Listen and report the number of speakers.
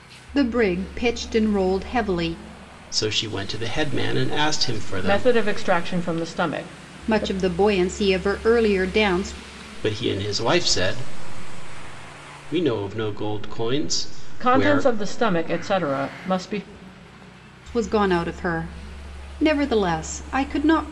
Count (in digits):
3